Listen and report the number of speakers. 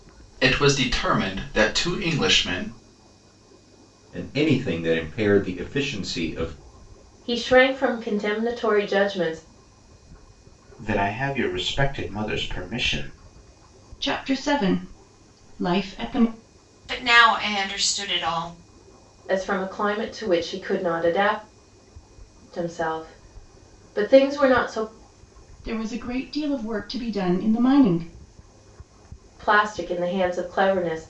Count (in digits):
6